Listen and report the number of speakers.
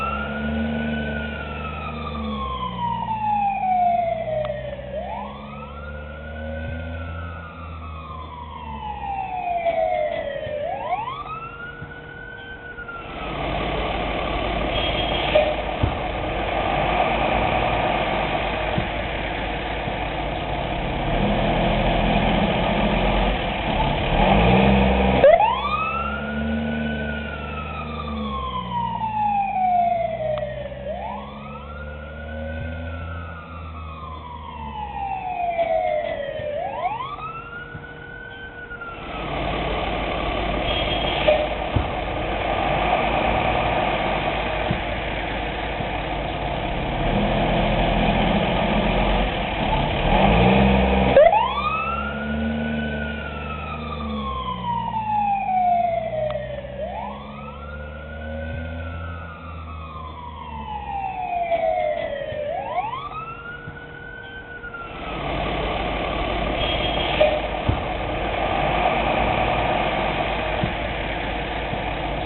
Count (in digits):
0